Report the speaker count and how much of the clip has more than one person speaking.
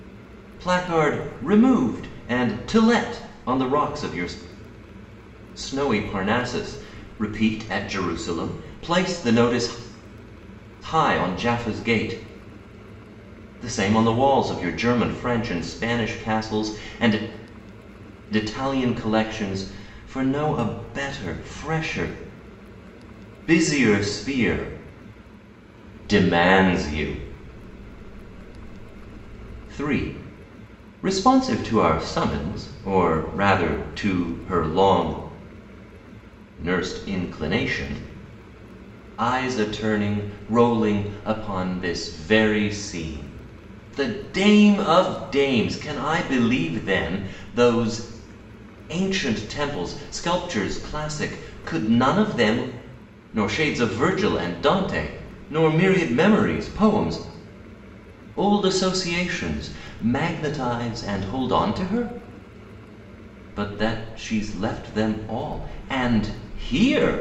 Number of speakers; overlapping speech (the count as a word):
one, no overlap